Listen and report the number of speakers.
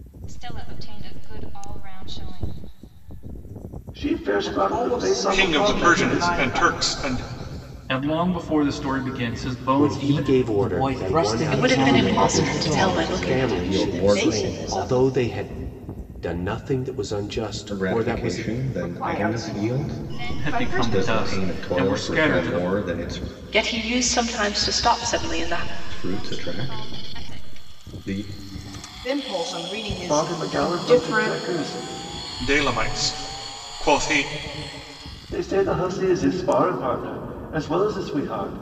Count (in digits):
9